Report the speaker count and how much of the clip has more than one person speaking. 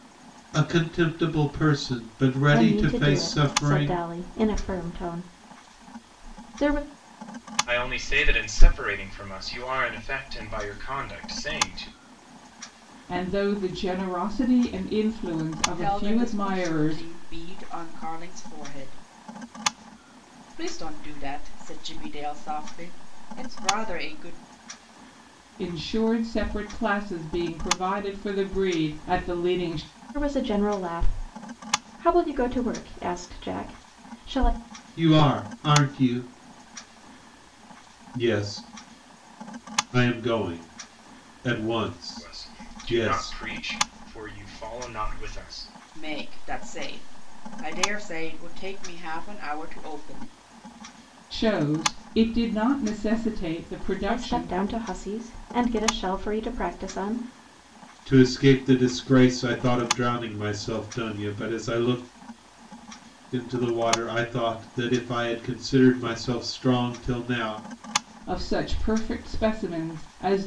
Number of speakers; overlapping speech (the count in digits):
5, about 6%